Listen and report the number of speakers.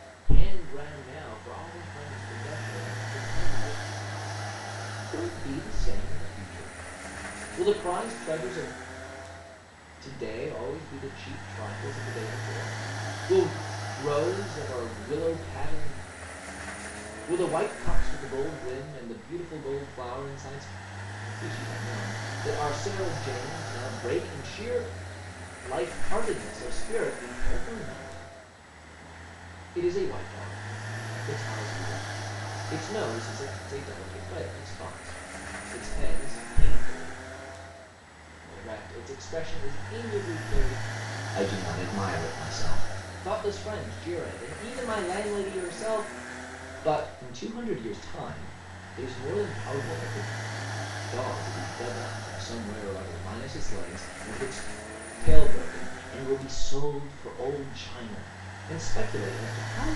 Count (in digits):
1